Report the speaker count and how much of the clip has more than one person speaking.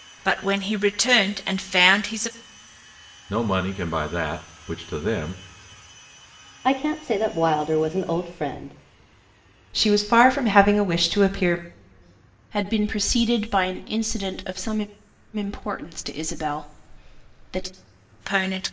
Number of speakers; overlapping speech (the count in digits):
5, no overlap